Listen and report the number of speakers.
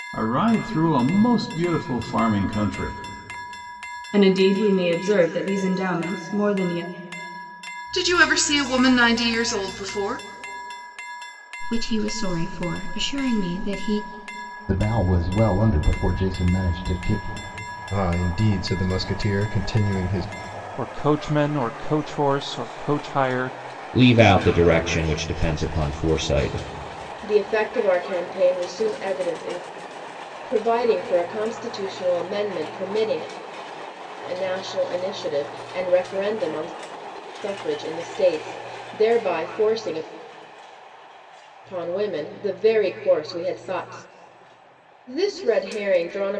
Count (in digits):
9